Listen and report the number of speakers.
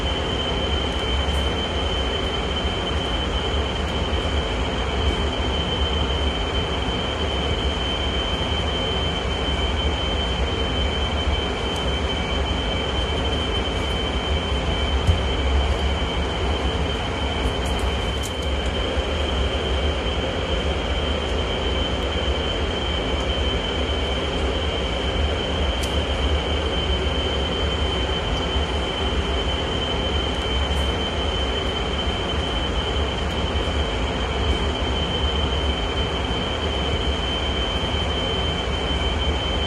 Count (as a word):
zero